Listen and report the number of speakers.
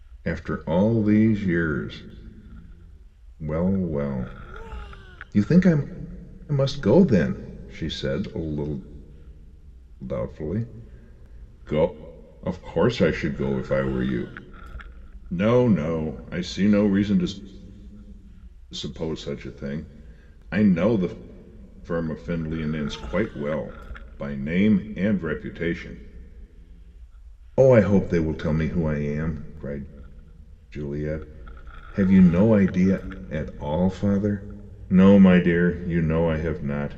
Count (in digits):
1